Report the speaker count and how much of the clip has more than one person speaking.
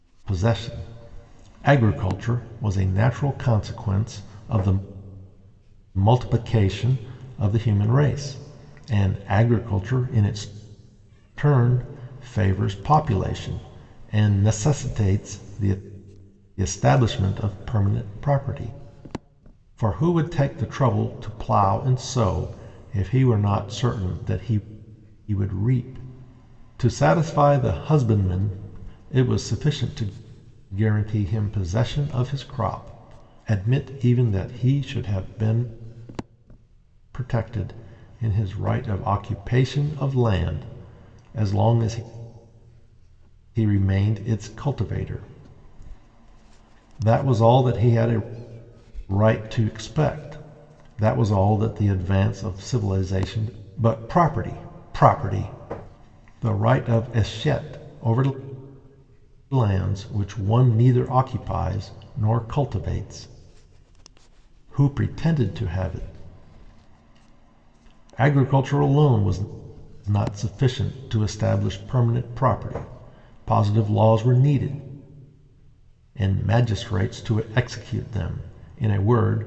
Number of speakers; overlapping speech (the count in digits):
1, no overlap